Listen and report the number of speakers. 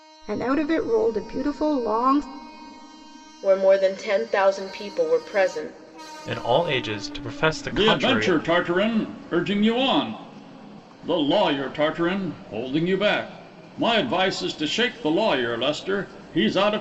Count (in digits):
4